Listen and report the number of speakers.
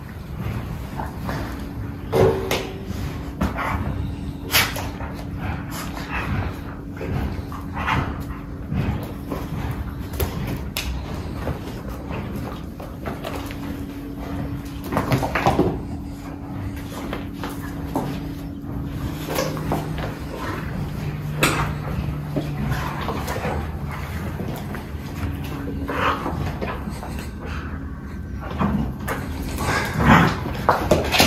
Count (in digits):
0